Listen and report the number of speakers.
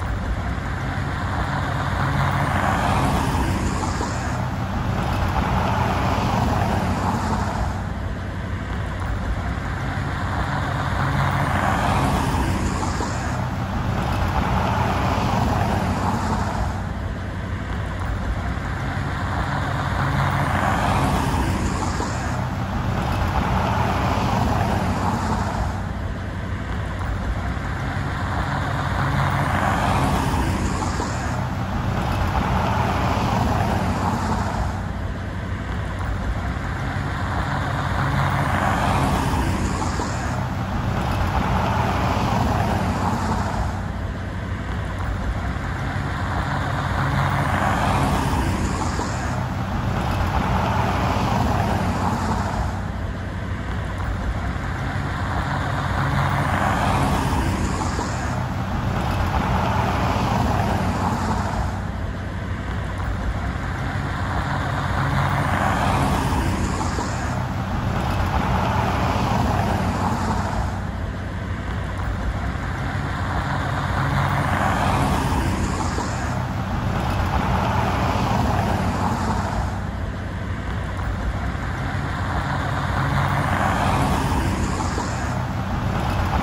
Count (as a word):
zero